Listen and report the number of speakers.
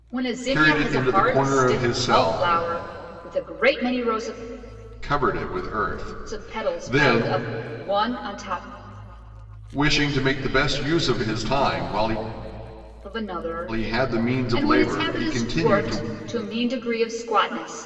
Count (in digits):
2